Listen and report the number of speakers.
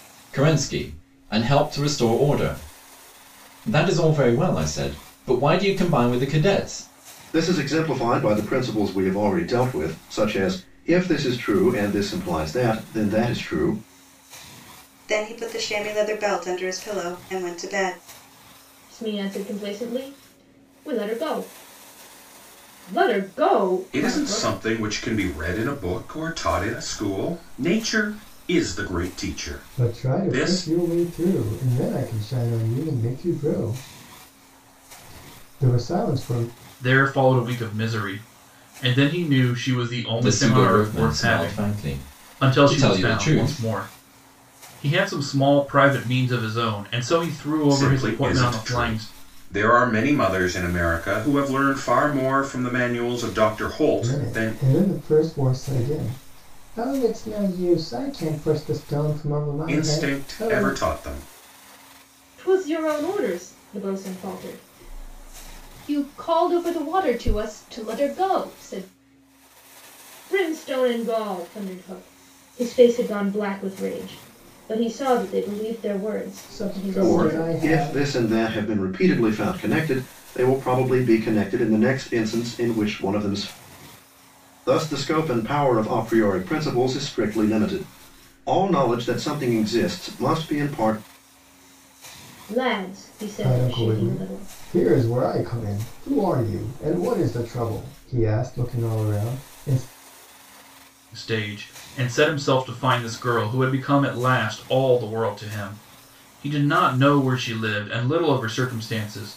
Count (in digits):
7